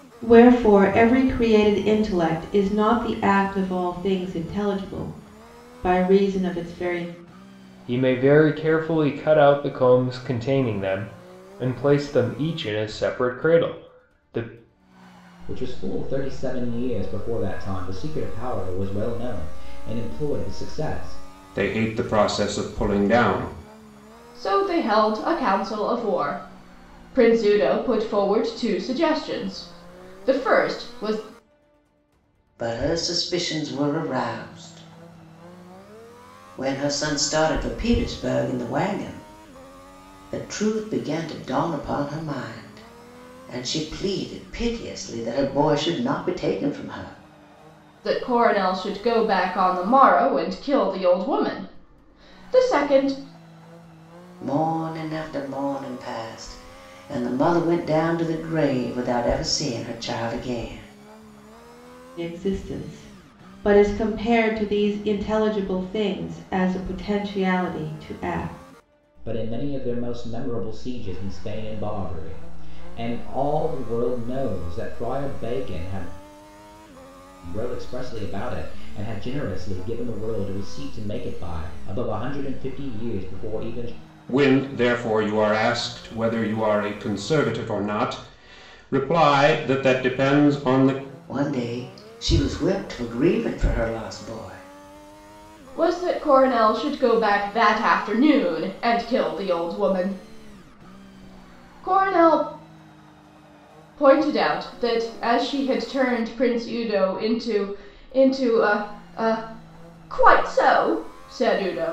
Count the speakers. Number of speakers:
six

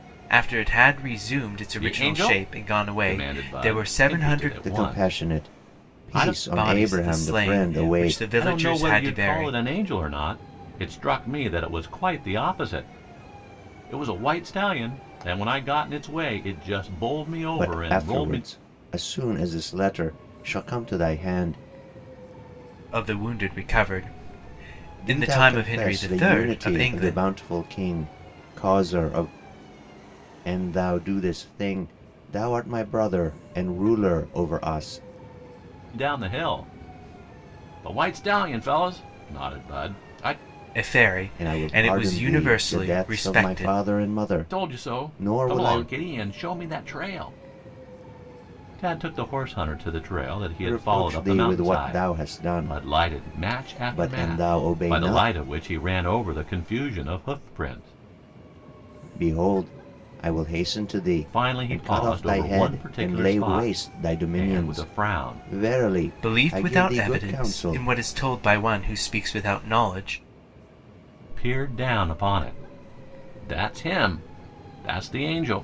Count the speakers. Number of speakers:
three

